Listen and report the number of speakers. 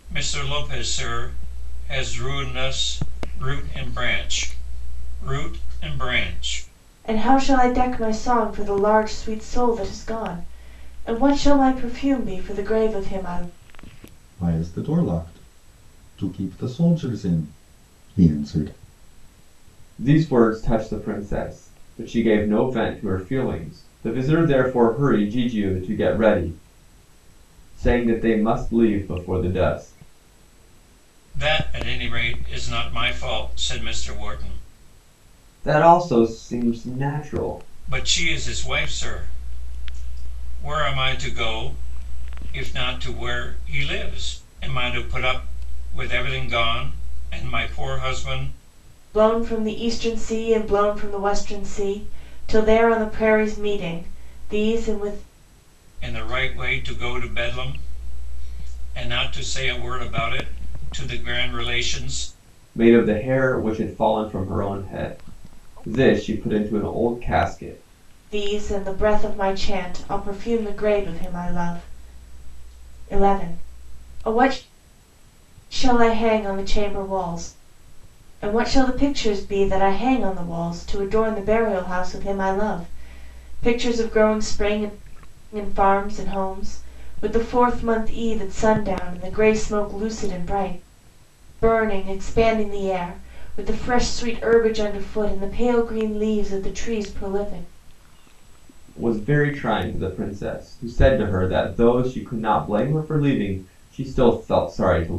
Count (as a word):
four